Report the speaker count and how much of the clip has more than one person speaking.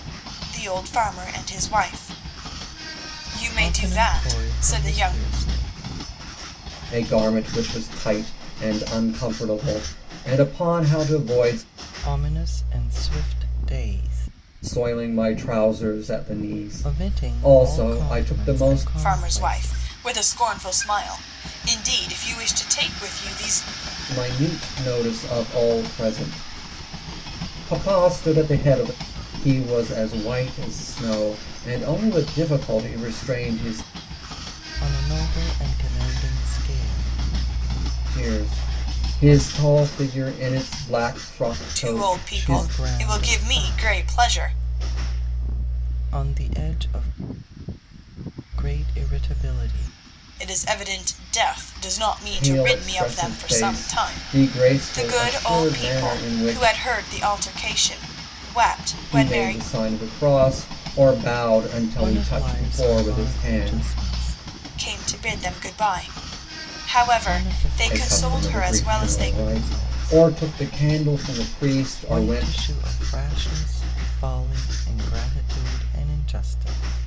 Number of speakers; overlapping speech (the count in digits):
3, about 25%